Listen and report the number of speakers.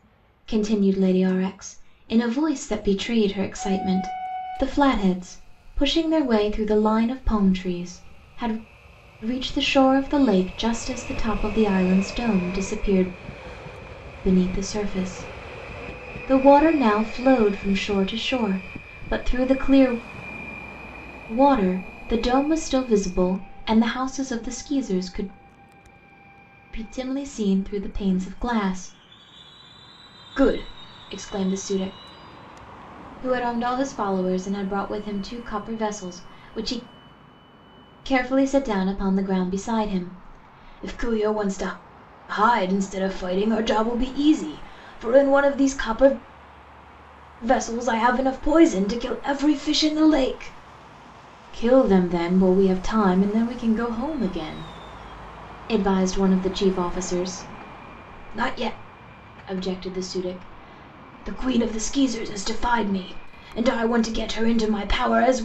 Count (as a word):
one